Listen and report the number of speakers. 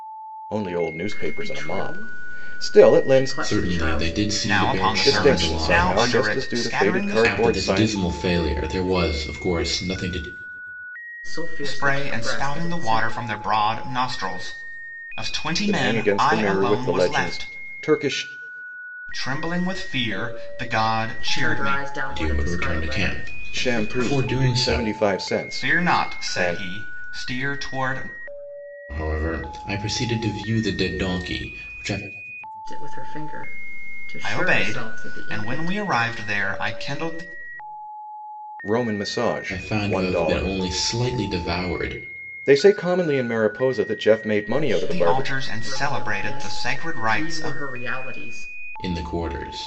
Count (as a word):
four